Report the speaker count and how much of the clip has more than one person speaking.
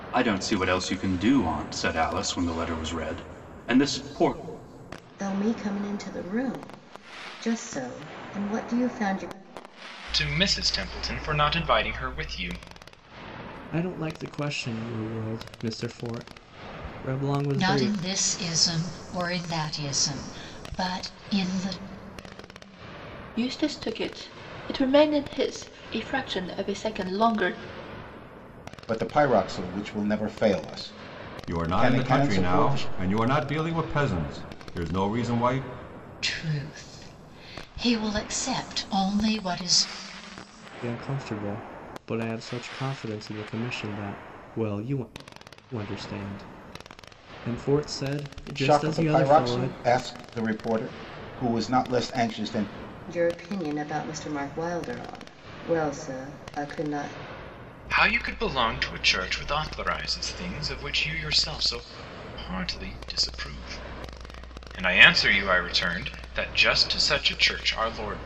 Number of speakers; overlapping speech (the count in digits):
8, about 5%